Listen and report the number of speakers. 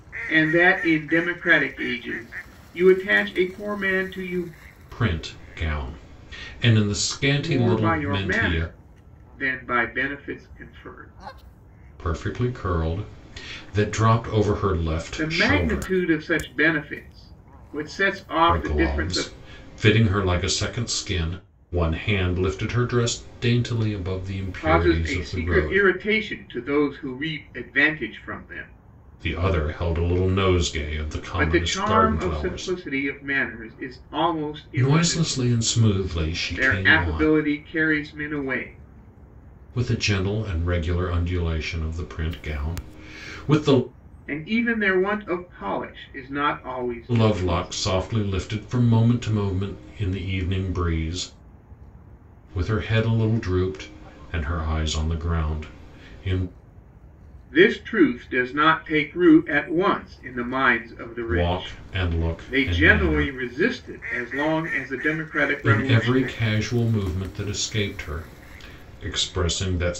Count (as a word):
two